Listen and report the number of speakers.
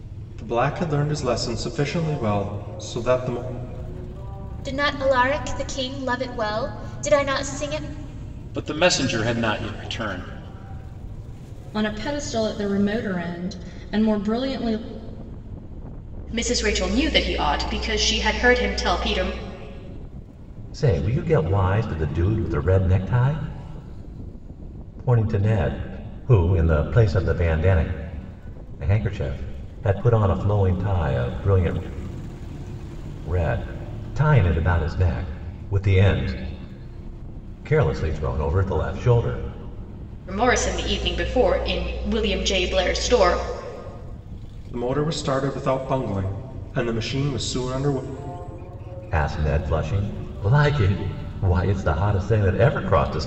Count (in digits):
6